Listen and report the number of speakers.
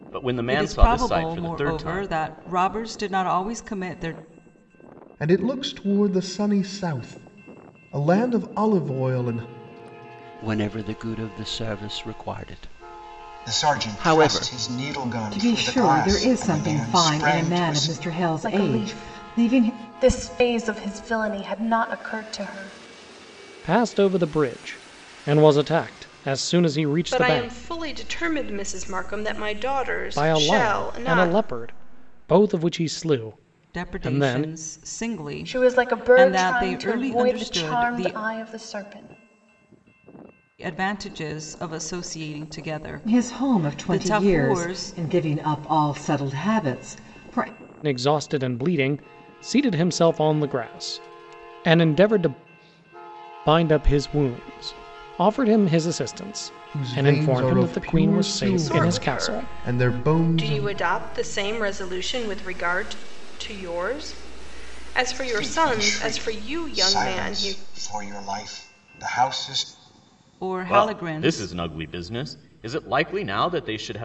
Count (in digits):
9